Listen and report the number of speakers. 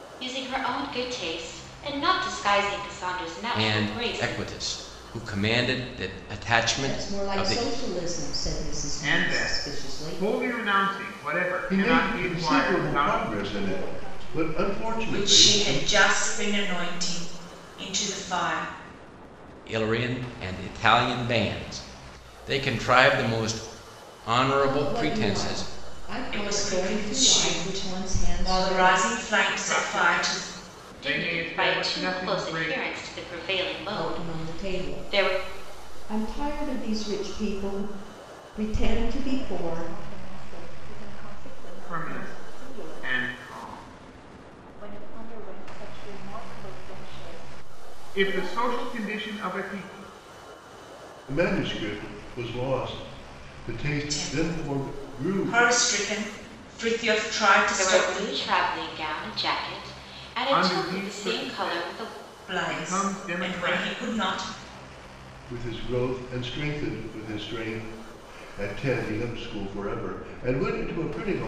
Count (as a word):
seven